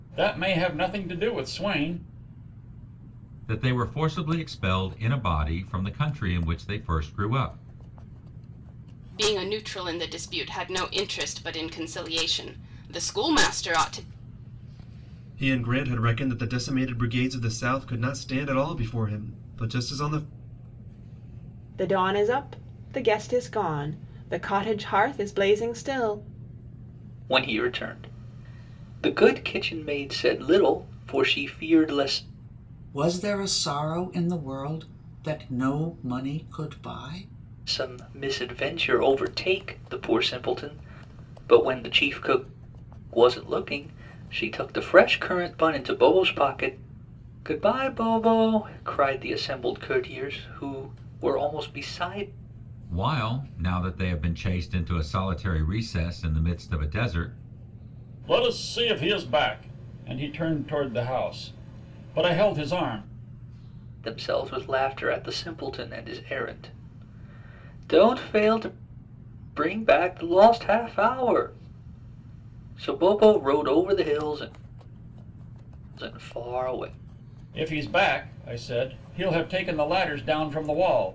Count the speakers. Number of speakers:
7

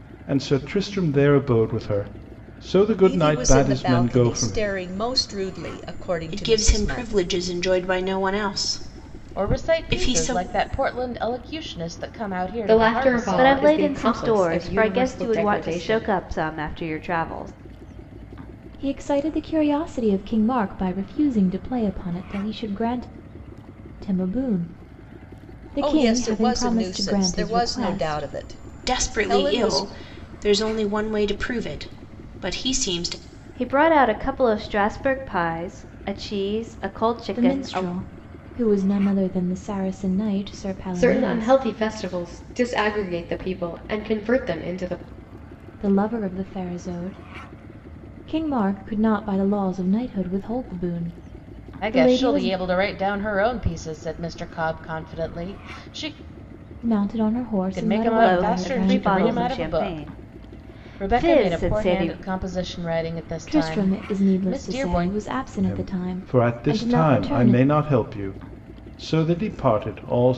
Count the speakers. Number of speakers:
7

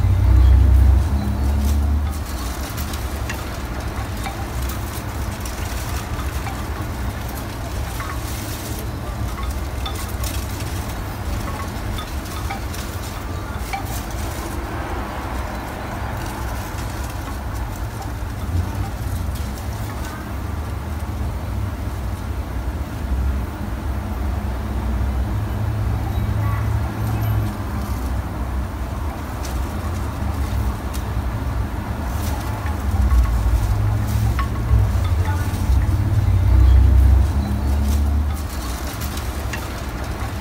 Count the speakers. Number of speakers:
0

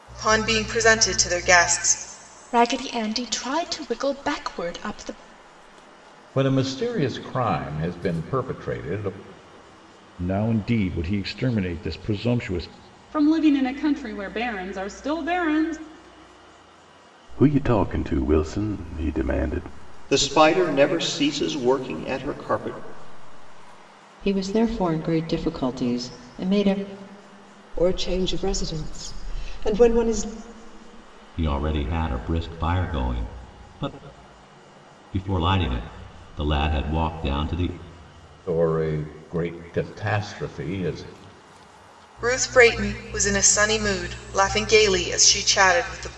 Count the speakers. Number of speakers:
10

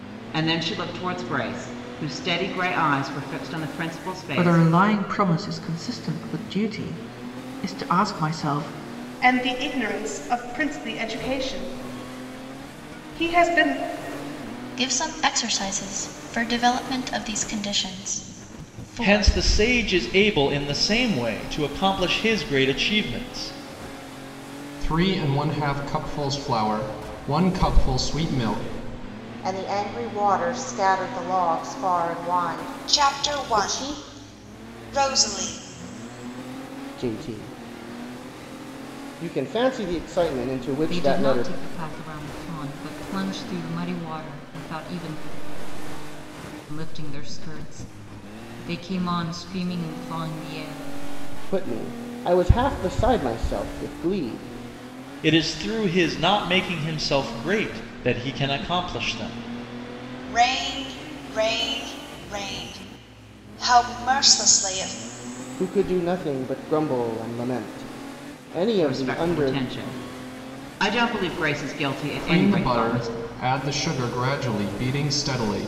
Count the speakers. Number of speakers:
10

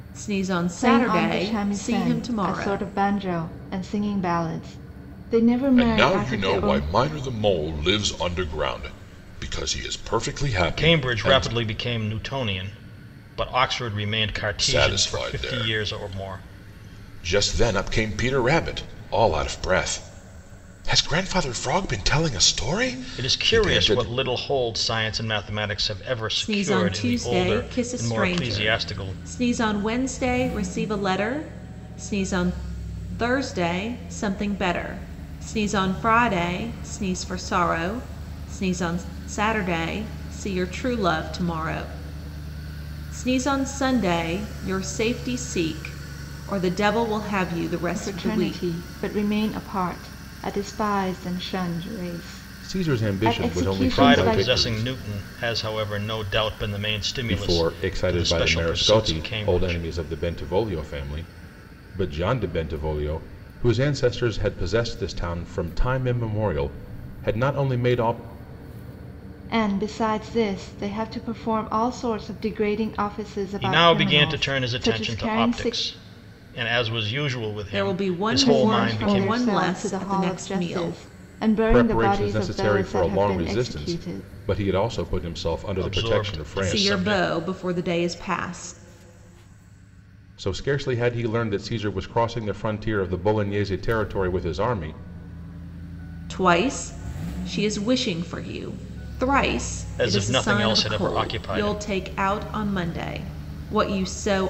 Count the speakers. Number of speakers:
4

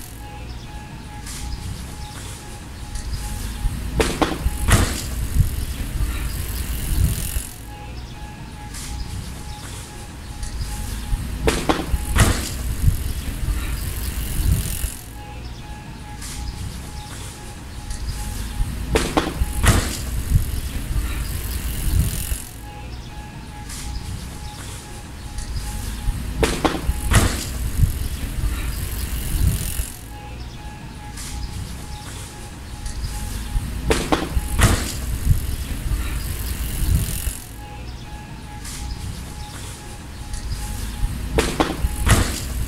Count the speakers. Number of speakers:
0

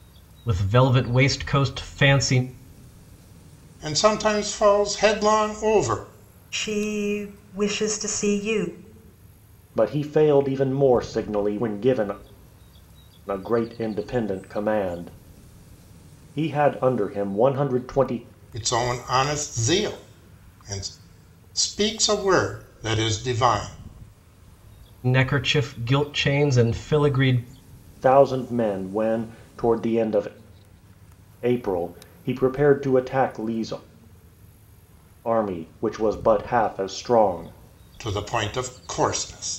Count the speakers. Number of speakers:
4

